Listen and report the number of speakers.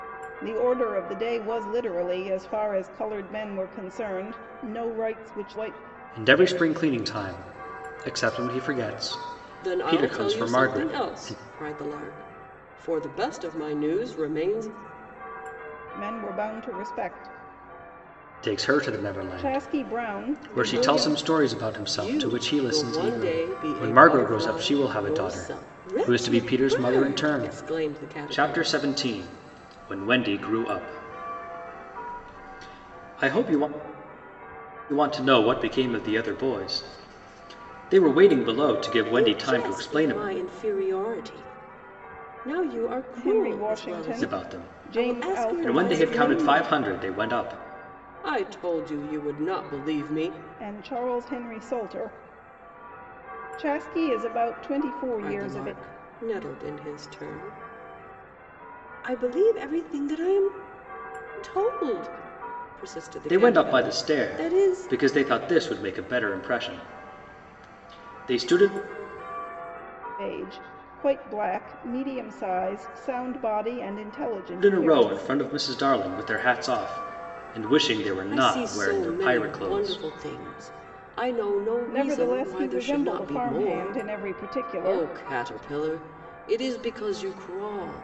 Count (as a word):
three